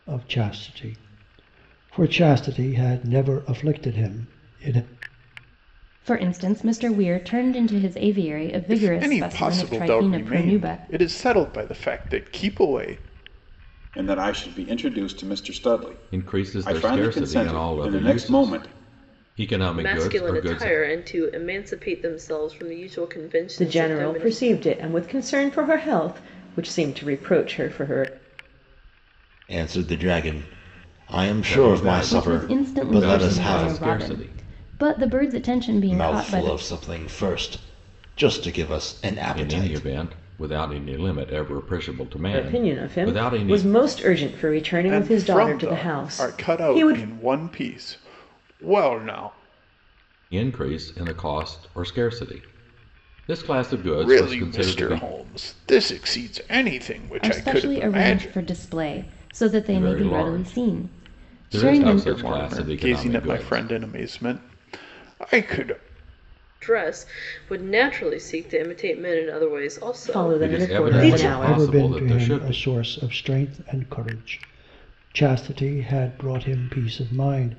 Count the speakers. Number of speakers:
eight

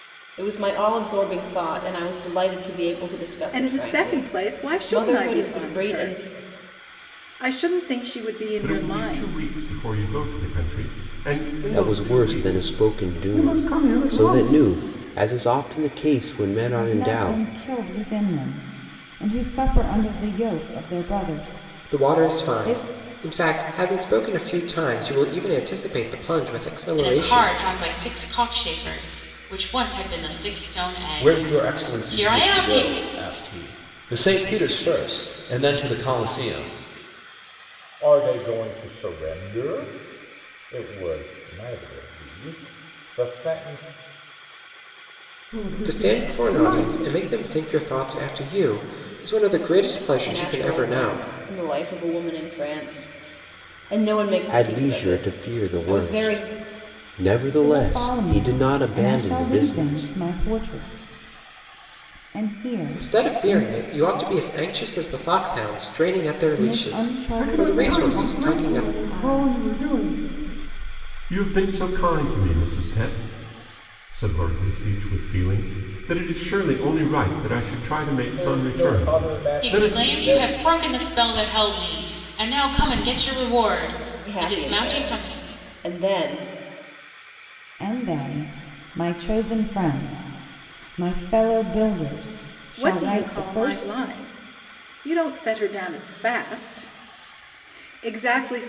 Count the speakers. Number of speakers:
nine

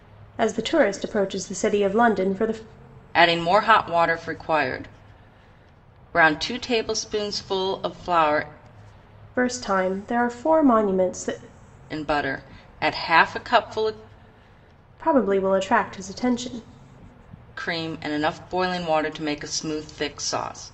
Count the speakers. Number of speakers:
two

